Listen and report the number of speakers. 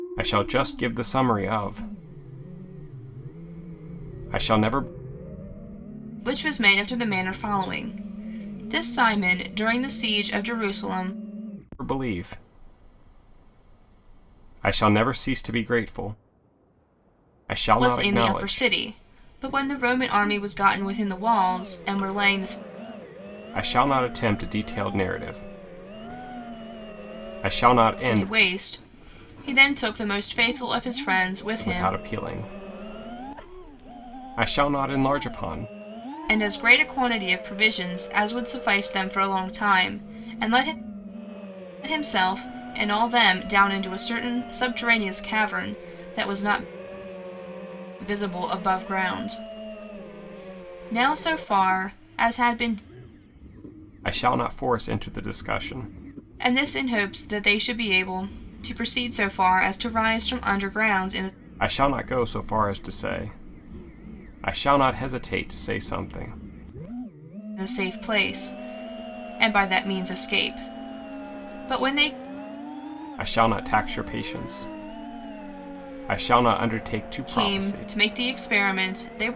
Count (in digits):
2